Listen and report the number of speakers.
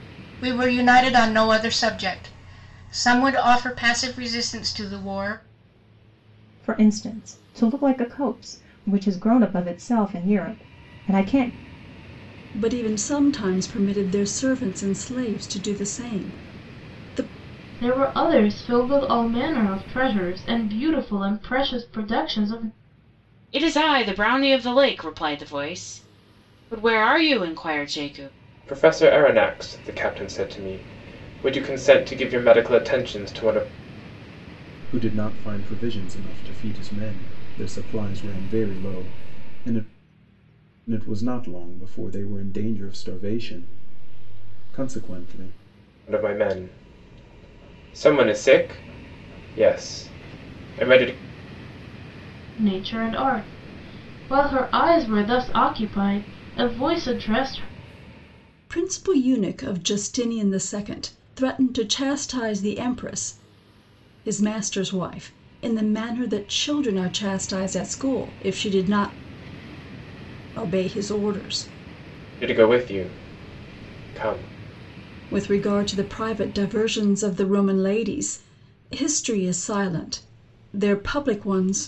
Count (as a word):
seven